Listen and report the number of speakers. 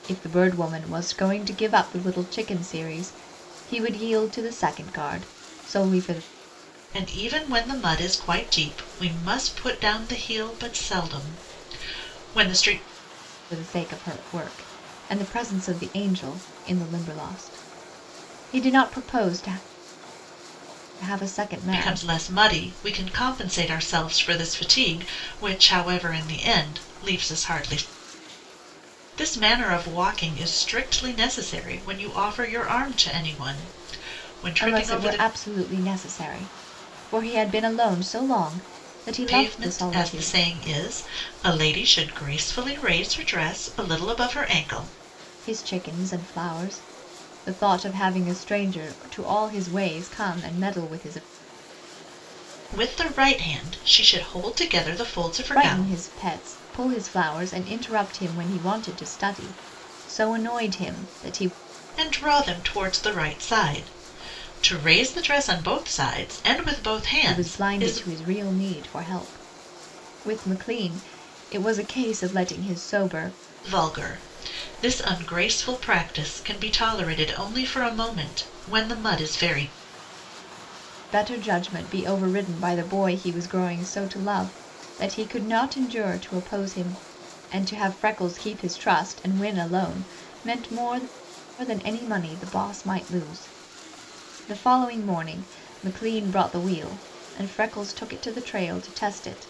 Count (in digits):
2